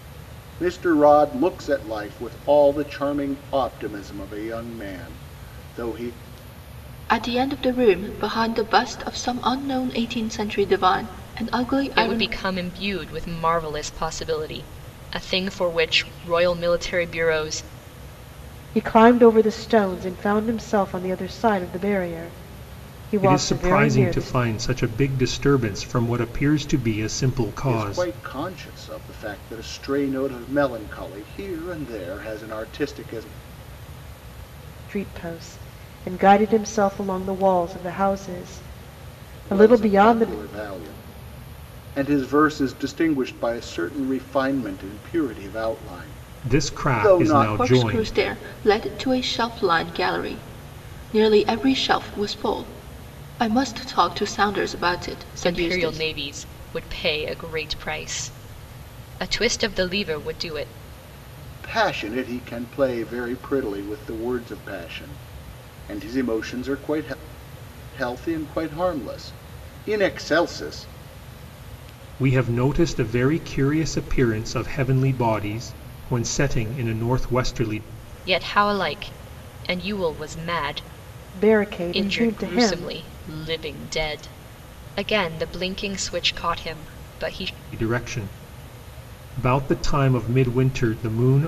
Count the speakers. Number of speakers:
5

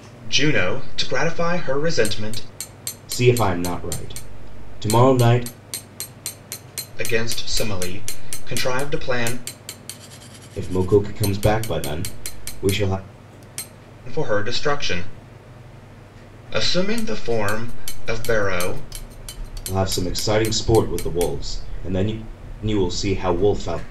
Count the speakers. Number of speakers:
2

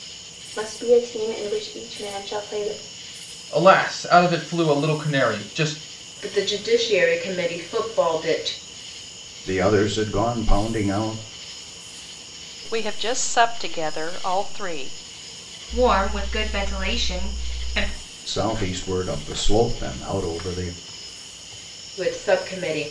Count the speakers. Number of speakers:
6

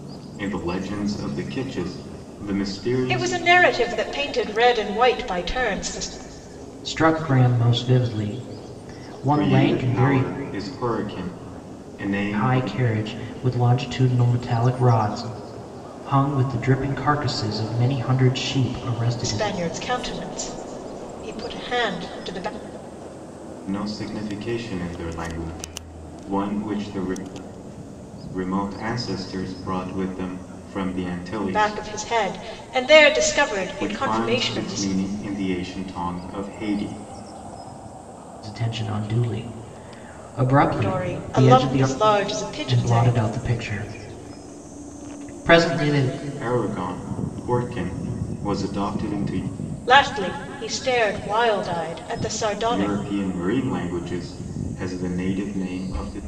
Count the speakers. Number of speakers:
3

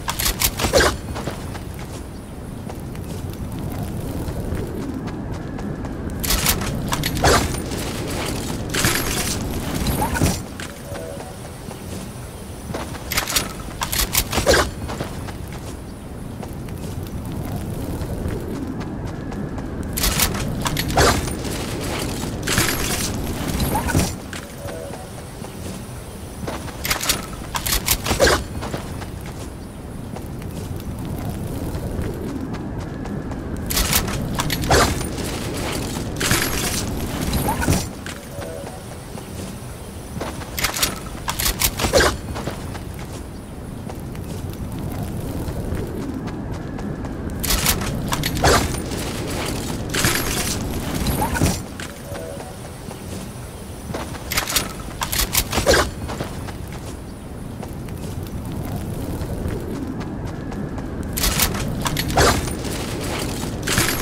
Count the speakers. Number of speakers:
0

